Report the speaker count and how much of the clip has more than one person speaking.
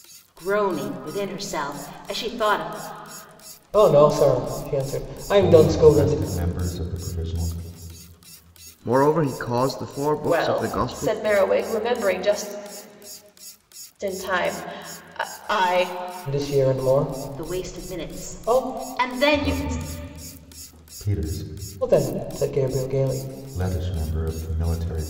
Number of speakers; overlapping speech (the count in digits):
5, about 15%